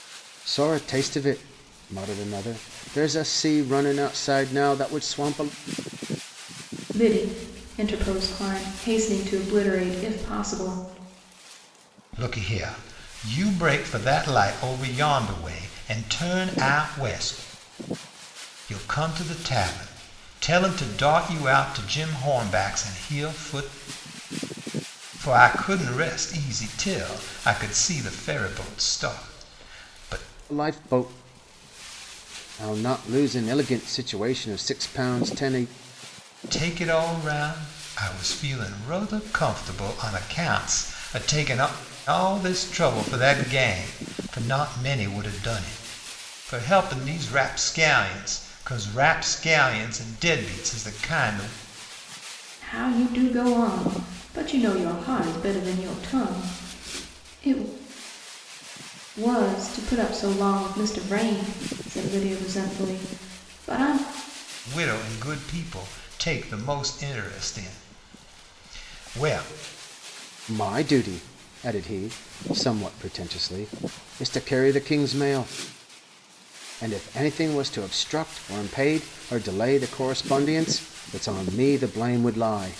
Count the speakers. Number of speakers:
three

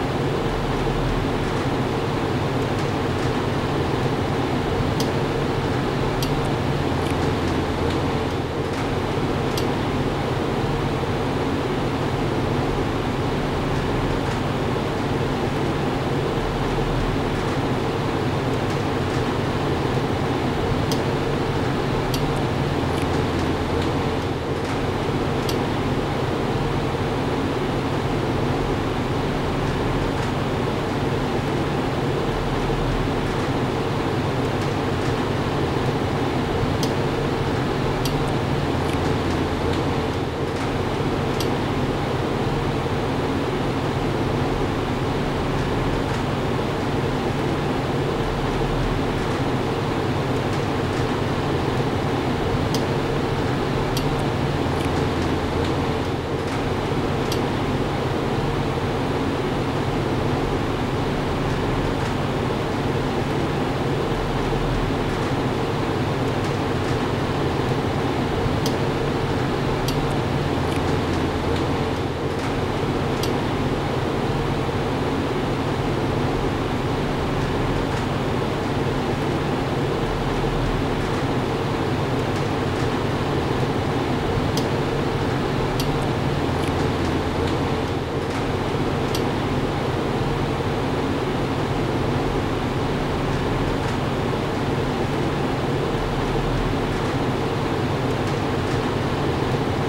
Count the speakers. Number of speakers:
zero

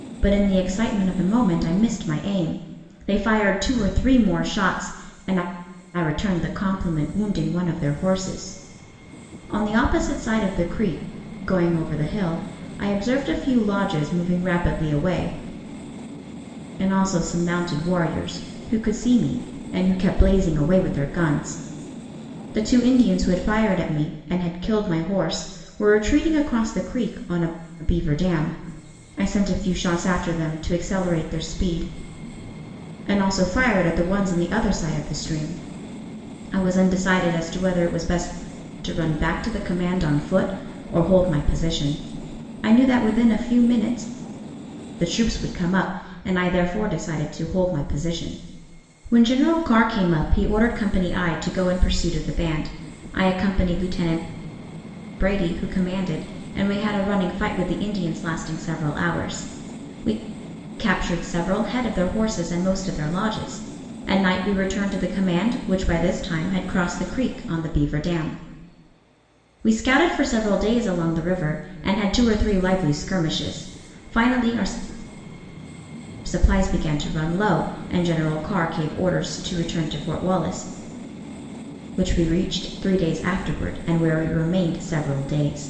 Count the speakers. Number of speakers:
one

